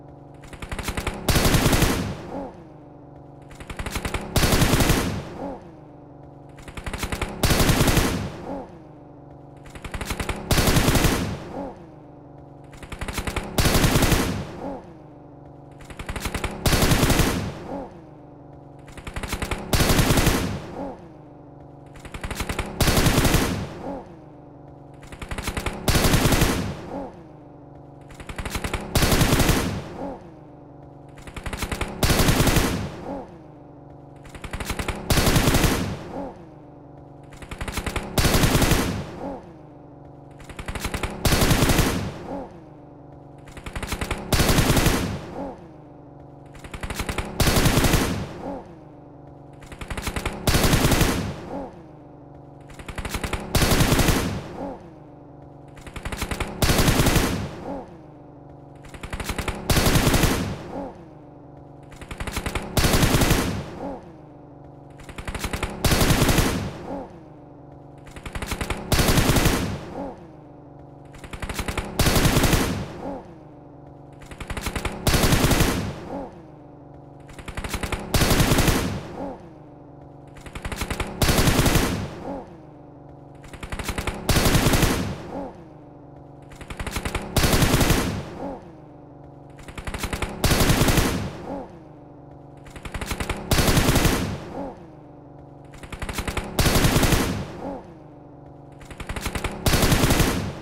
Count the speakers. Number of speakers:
zero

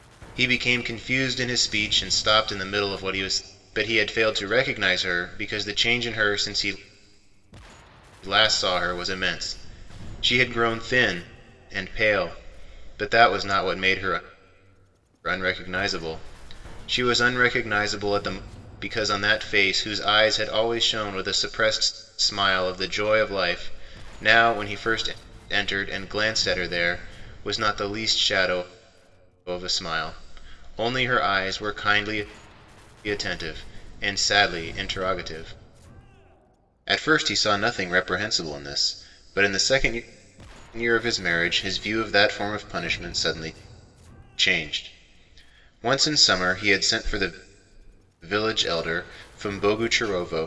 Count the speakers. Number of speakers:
one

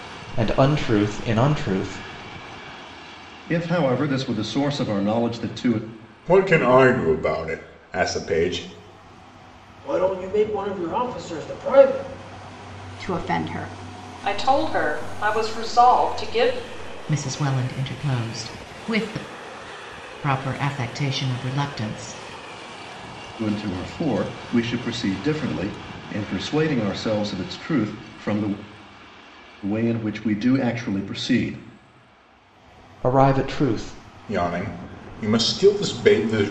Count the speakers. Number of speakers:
seven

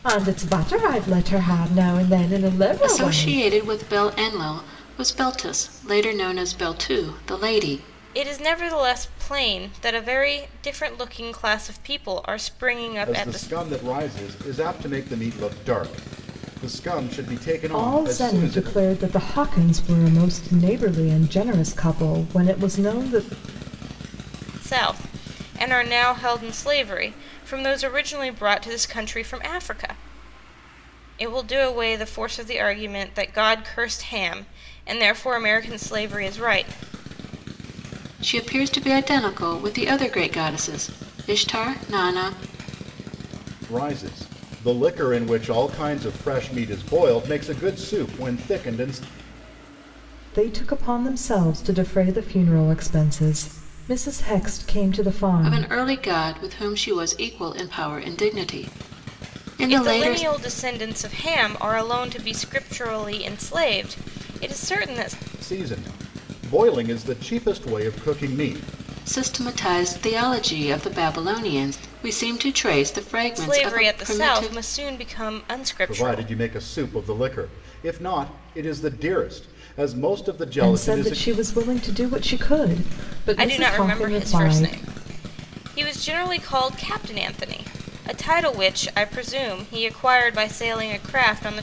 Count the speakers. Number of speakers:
four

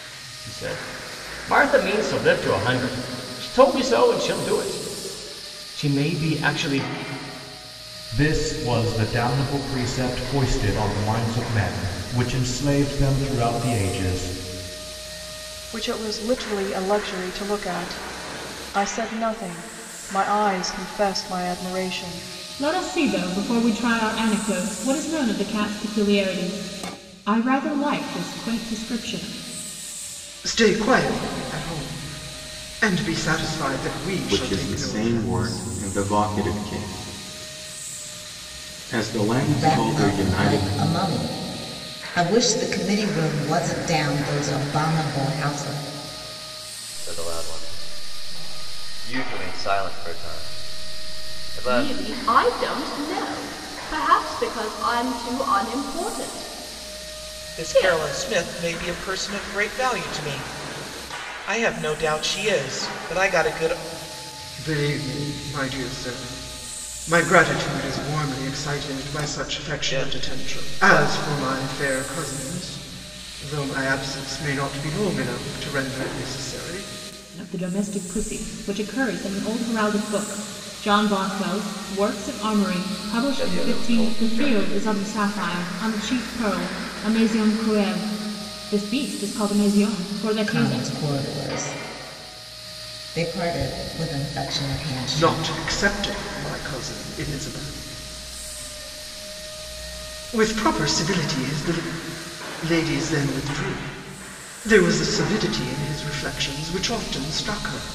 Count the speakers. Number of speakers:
ten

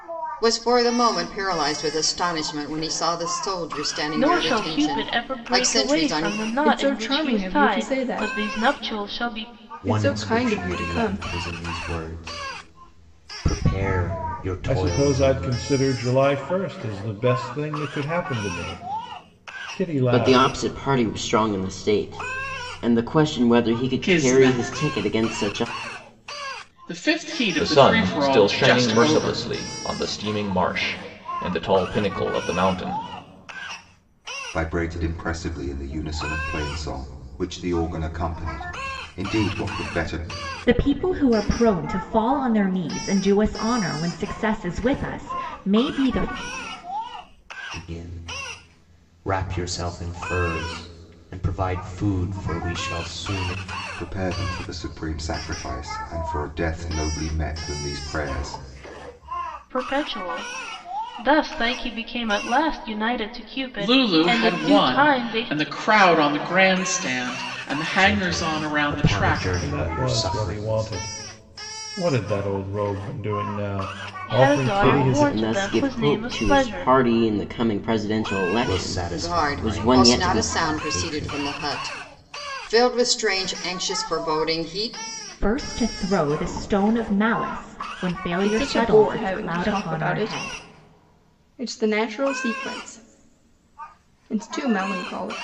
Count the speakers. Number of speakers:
ten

